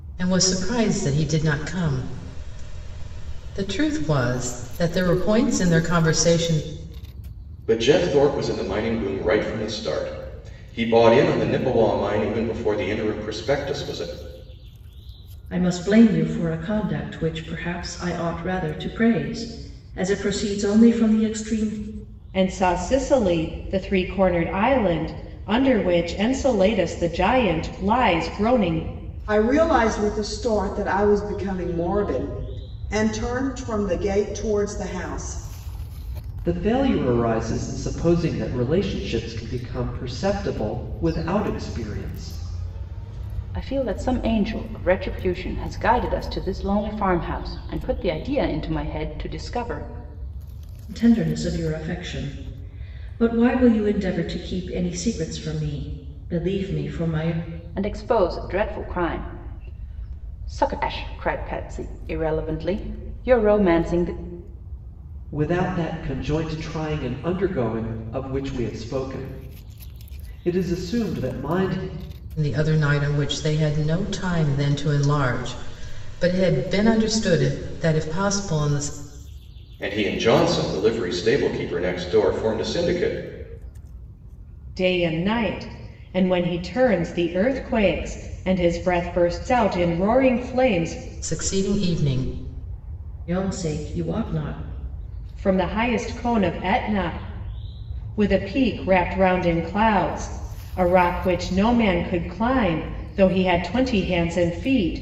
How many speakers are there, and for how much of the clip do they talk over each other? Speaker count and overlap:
seven, no overlap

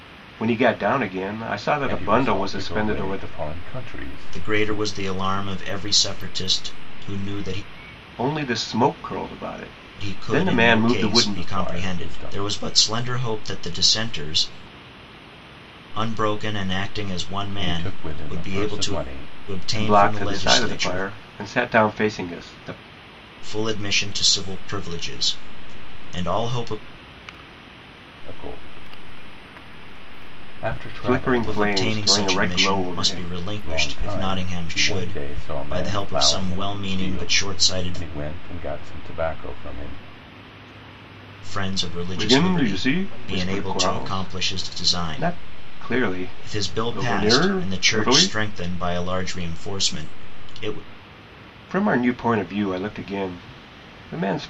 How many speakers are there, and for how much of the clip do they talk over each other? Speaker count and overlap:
three, about 37%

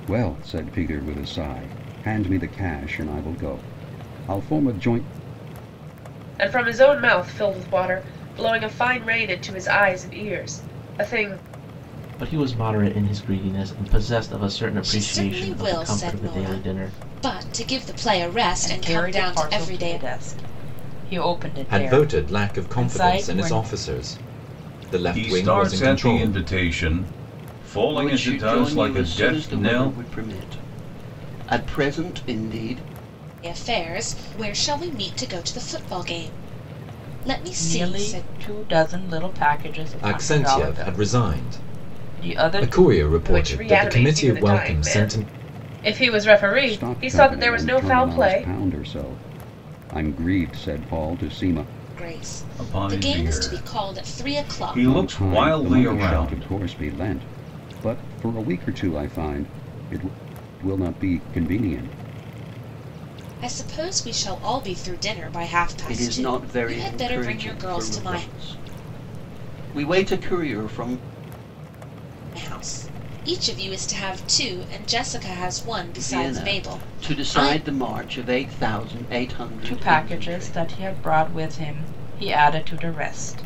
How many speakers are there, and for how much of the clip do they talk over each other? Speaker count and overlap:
eight, about 30%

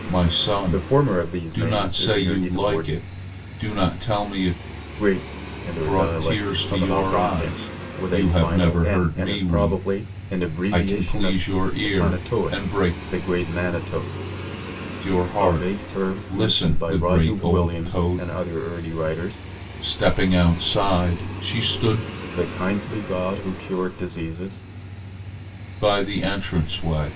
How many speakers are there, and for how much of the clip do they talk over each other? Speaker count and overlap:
two, about 41%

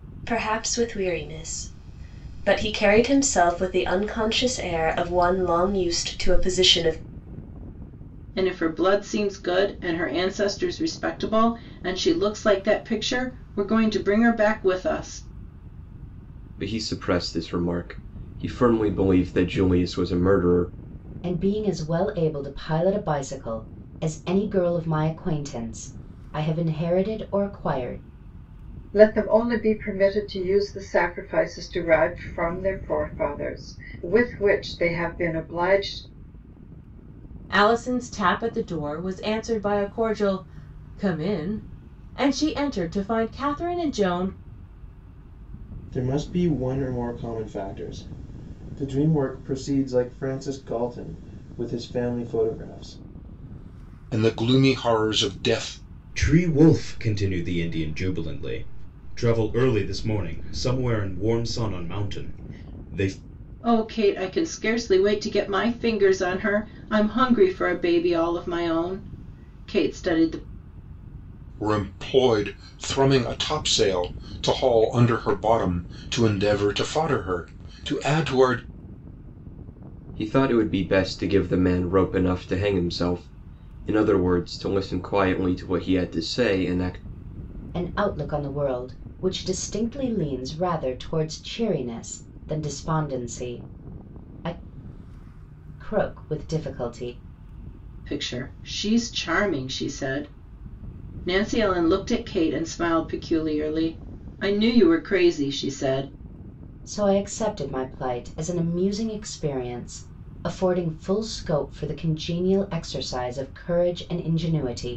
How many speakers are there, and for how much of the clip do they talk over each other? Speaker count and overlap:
nine, no overlap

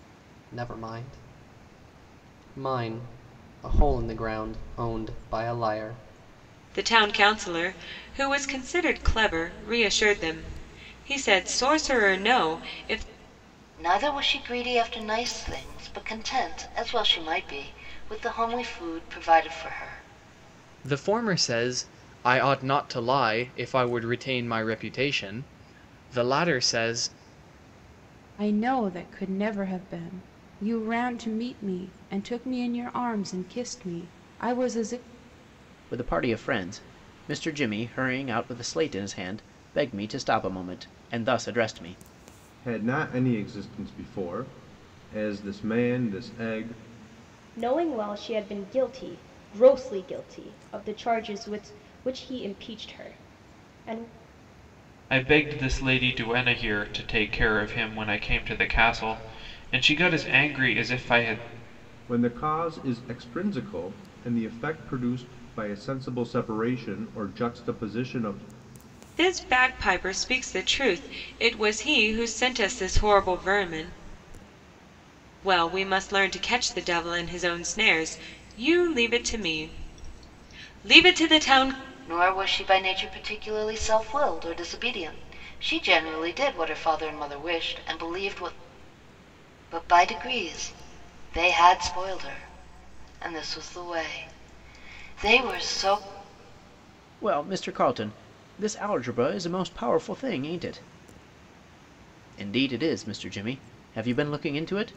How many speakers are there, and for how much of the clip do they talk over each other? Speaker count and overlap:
nine, no overlap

